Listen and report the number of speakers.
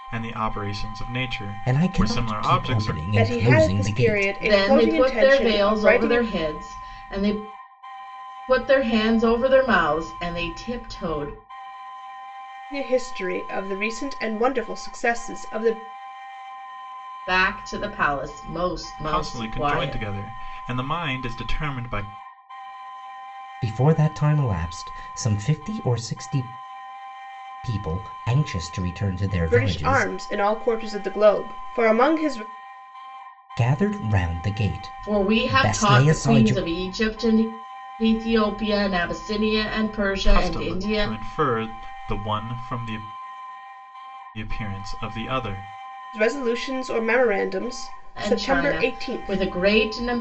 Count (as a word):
four